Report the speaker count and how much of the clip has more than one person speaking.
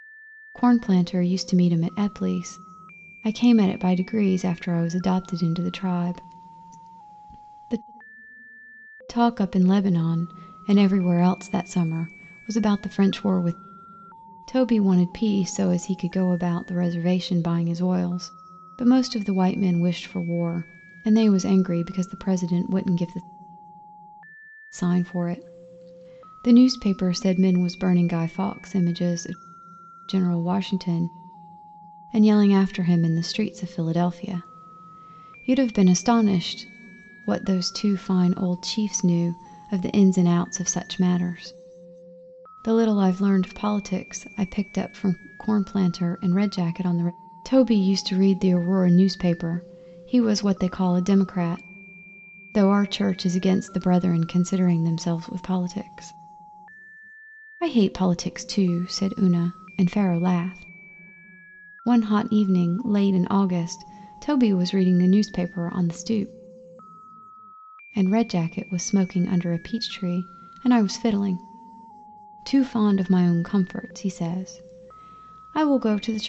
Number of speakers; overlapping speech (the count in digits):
1, no overlap